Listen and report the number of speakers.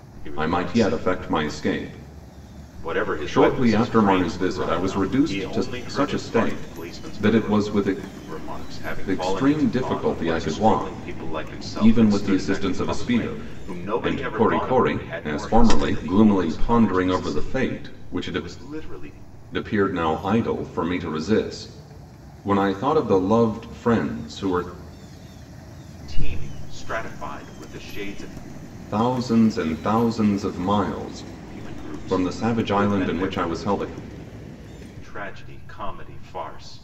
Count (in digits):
2